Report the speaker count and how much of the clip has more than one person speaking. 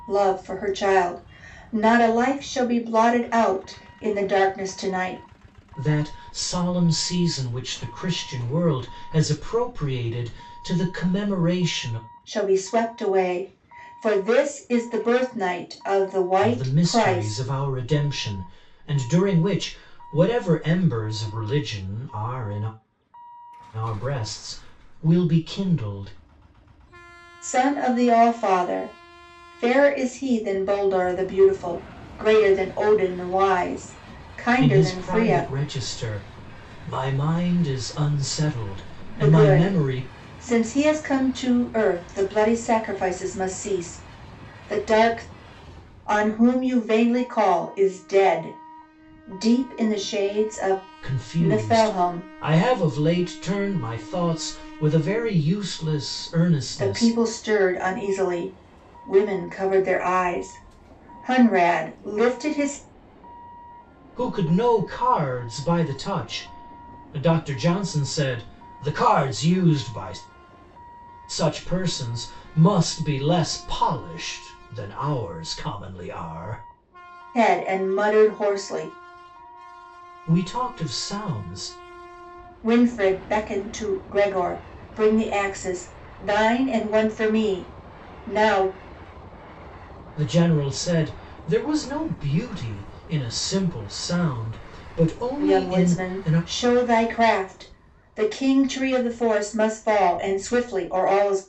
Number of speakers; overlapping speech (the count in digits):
2, about 6%